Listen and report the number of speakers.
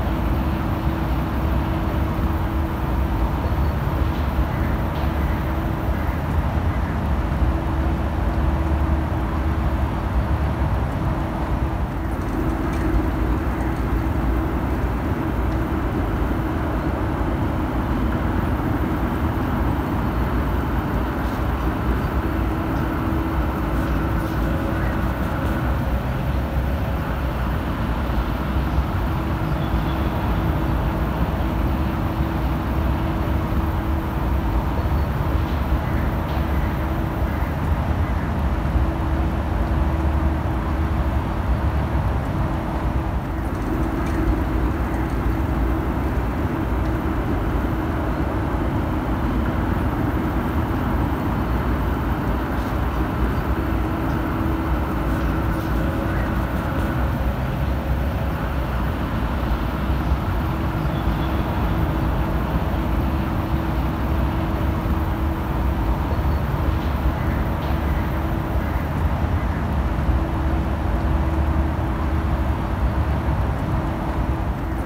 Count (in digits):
0